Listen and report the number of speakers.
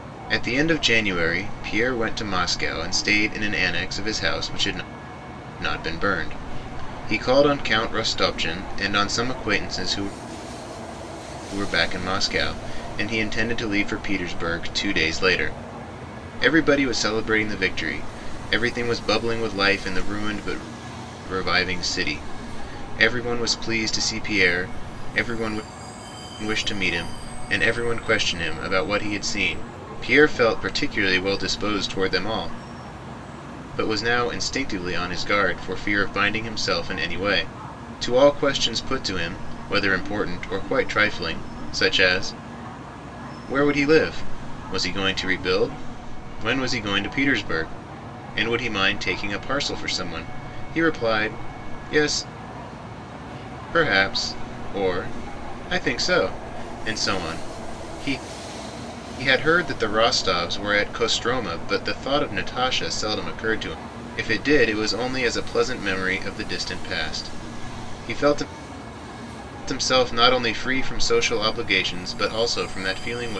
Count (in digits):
1